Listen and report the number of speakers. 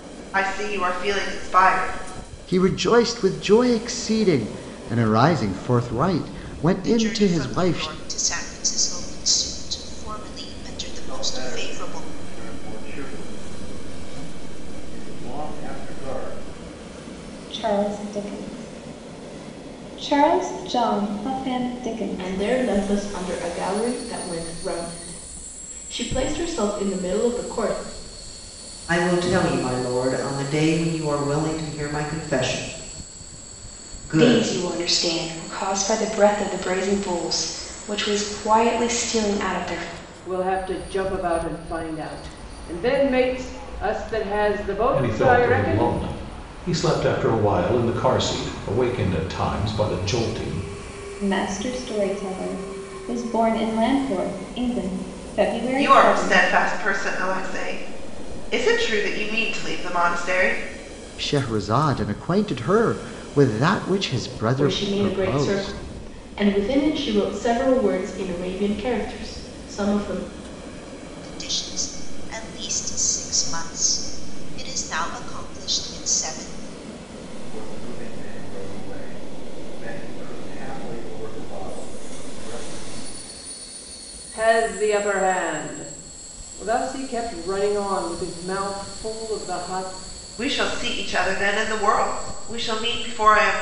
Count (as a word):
ten